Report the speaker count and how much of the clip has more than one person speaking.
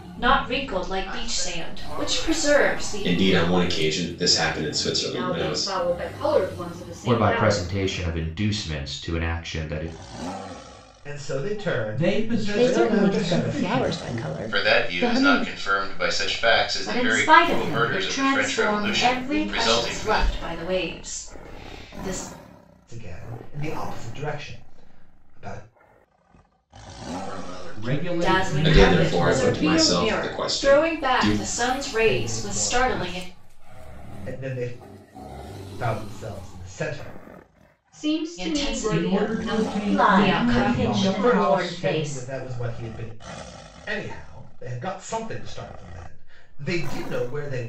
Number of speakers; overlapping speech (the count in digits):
10, about 41%